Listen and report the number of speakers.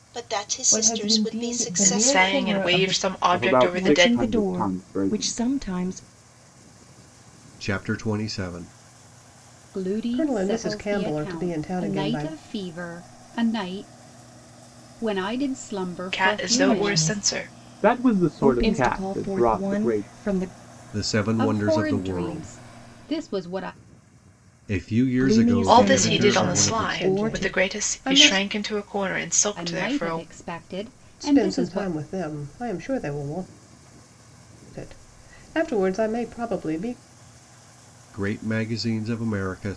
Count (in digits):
8